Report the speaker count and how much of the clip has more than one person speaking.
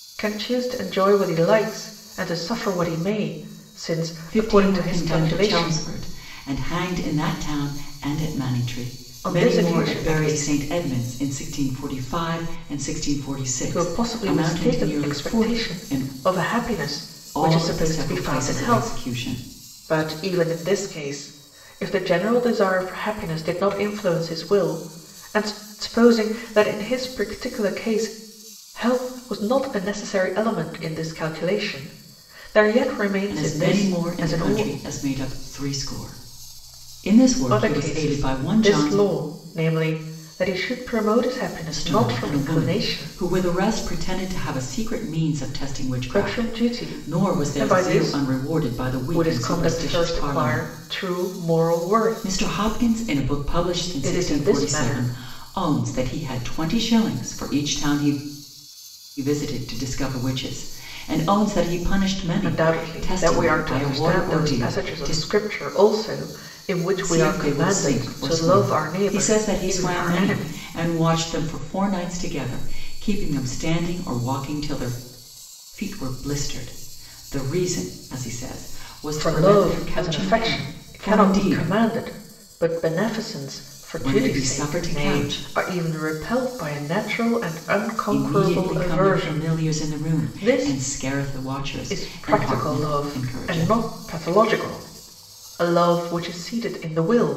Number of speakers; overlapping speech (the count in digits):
2, about 34%